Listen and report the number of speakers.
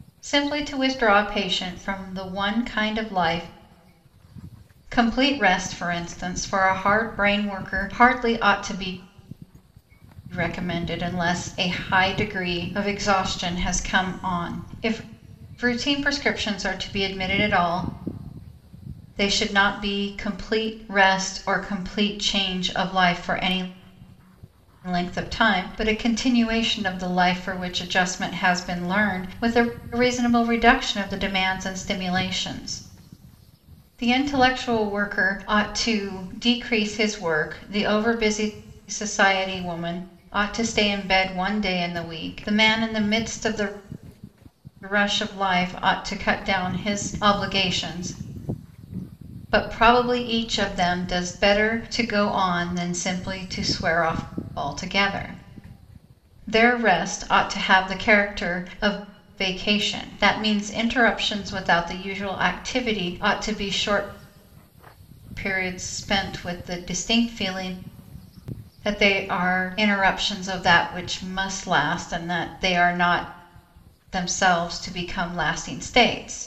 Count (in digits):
1